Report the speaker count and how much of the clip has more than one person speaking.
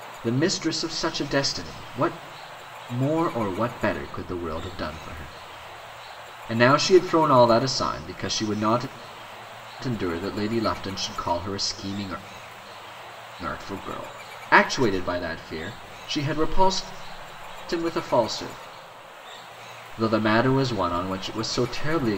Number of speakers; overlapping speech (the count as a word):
one, no overlap